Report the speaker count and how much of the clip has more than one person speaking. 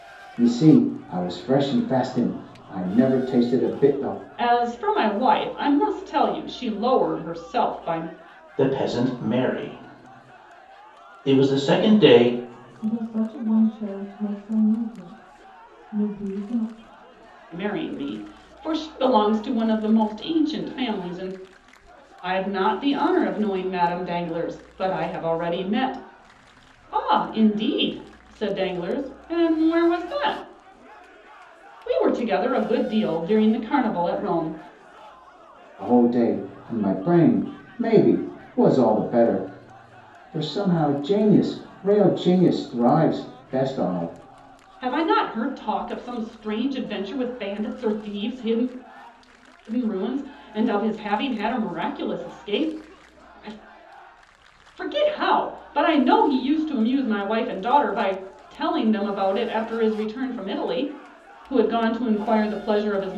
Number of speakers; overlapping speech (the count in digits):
4, no overlap